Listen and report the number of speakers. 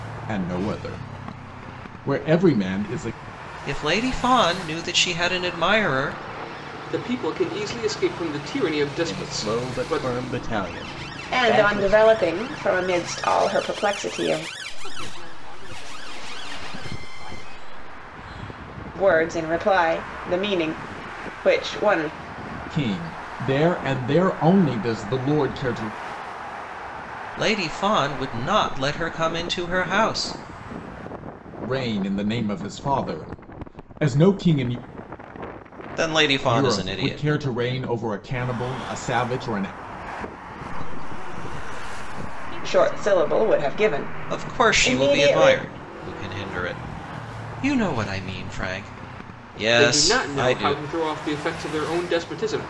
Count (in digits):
6